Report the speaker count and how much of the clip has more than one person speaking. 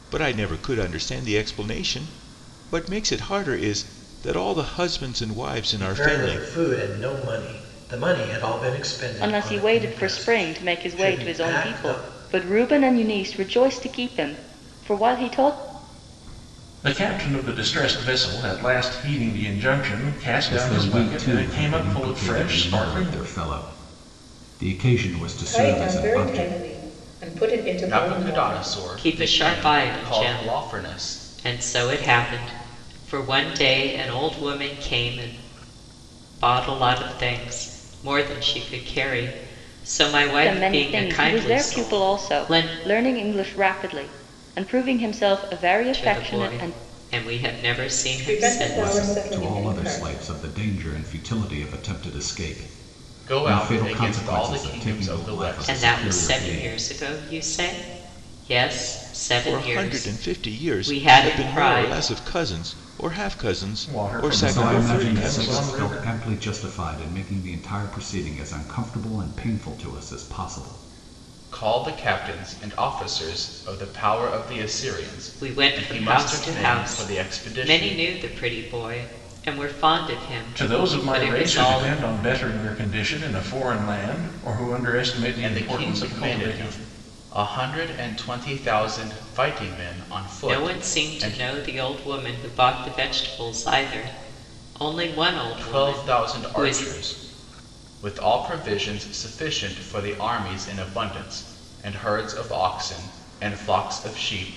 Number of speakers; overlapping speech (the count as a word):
eight, about 31%